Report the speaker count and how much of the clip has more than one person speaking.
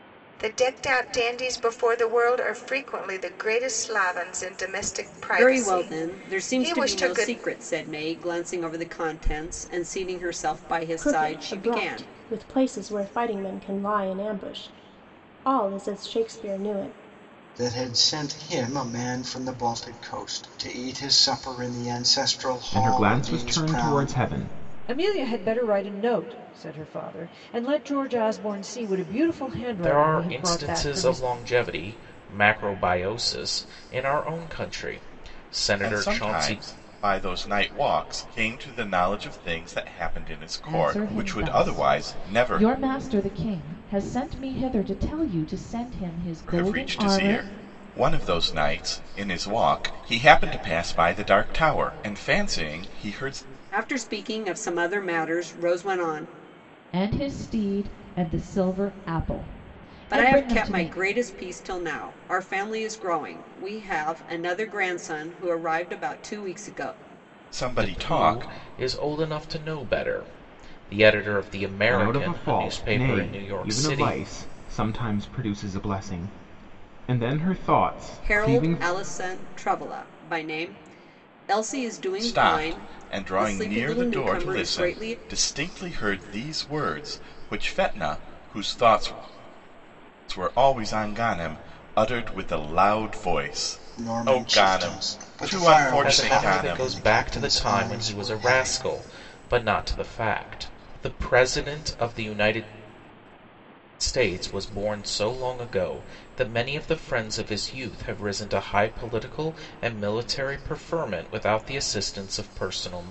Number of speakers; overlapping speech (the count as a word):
nine, about 20%